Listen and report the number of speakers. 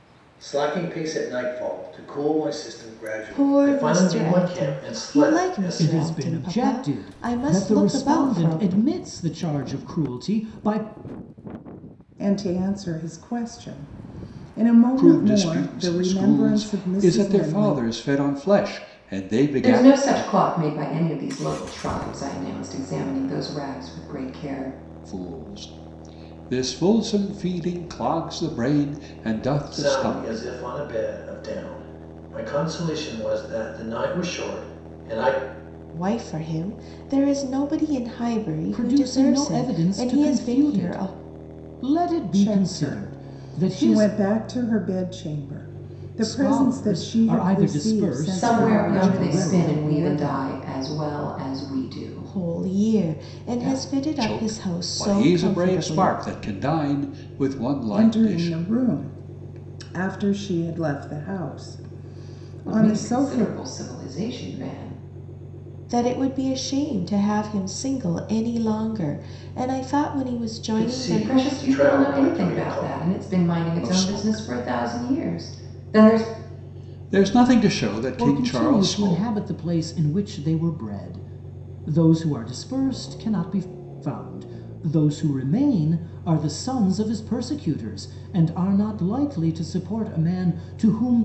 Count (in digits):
6